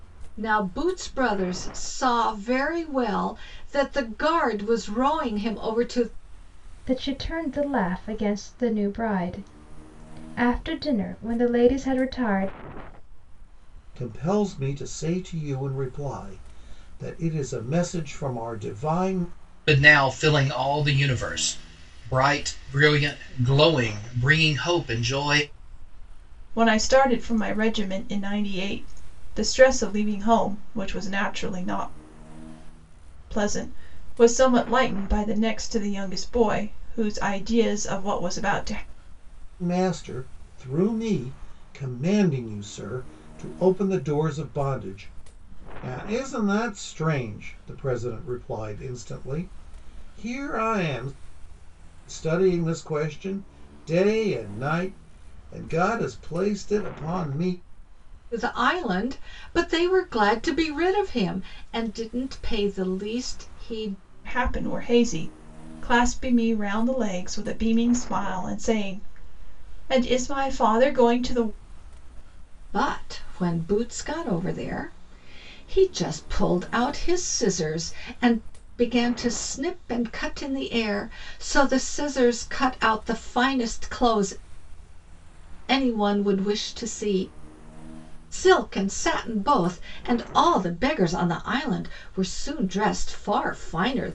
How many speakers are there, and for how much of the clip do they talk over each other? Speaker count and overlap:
5, no overlap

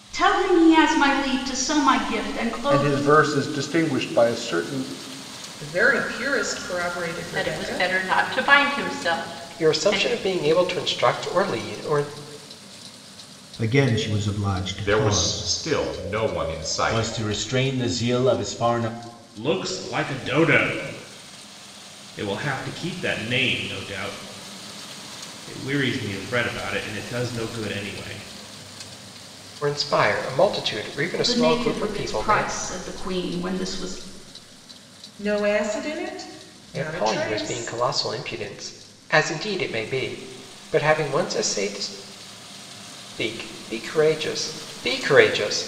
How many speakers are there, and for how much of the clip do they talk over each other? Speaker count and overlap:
9, about 10%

